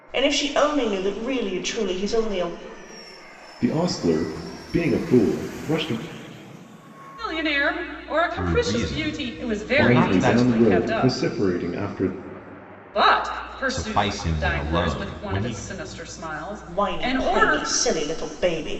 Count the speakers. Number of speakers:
4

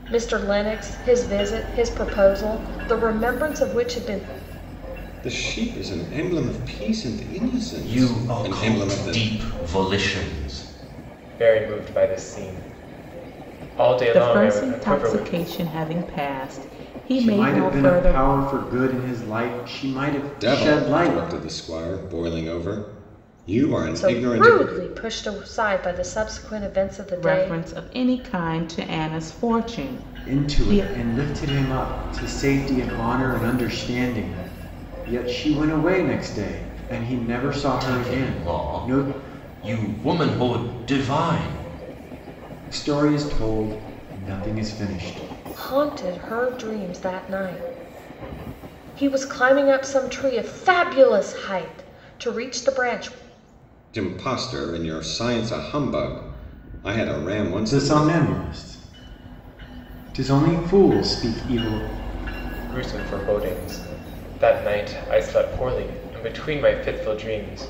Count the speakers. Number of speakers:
6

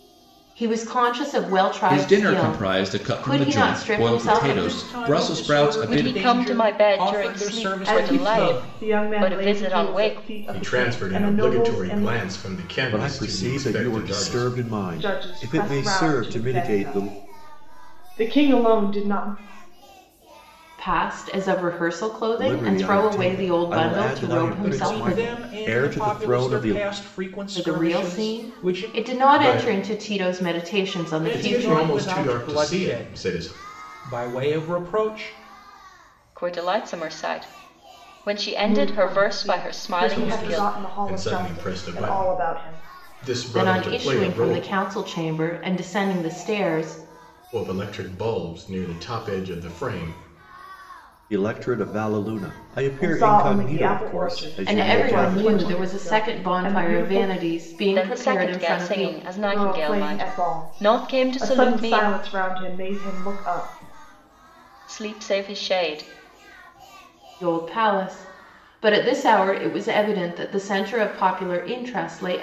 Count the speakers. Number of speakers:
7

